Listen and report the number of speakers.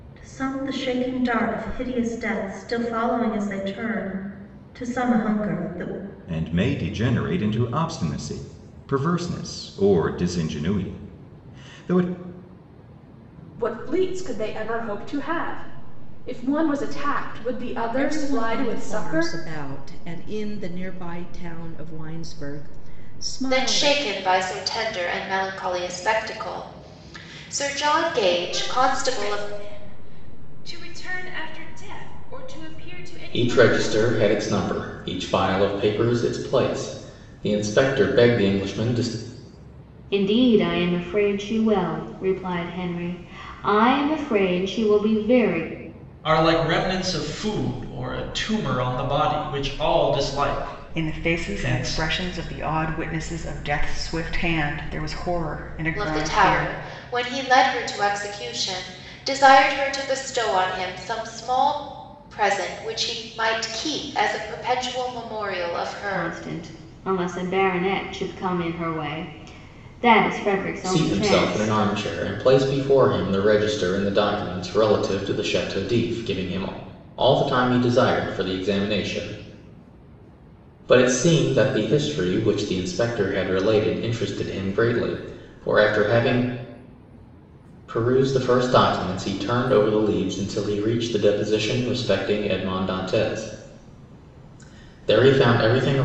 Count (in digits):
10